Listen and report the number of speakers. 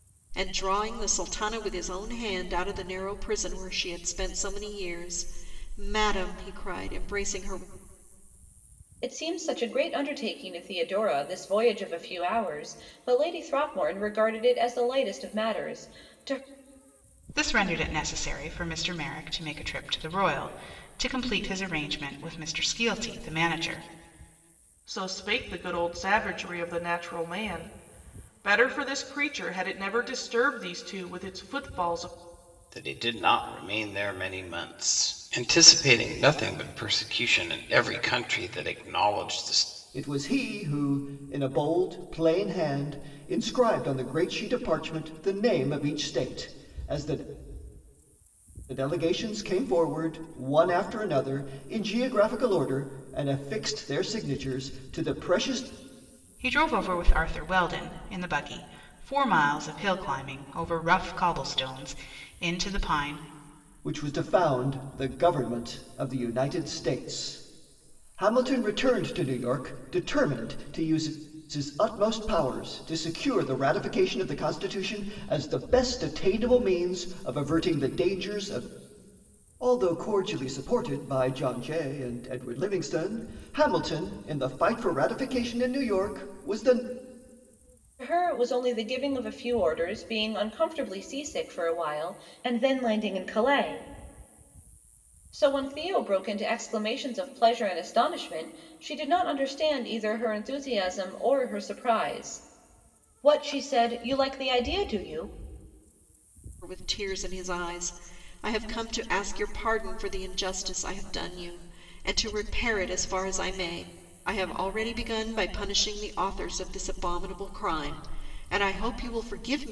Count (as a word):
six